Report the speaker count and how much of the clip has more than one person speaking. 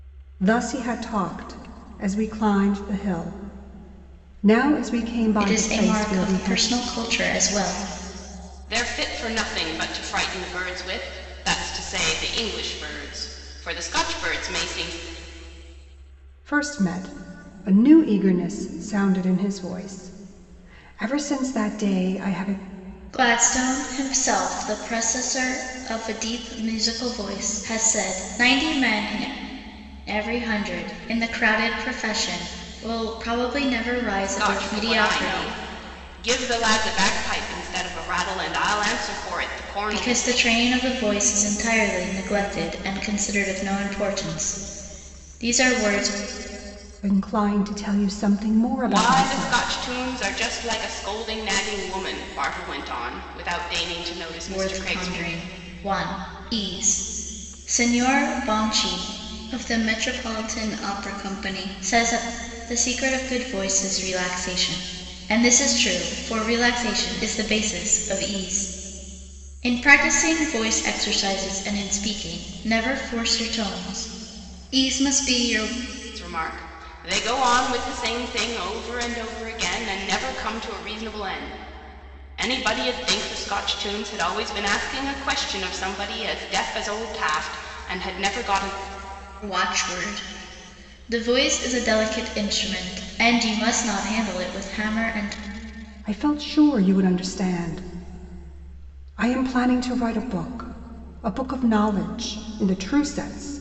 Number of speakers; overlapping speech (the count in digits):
3, about 5%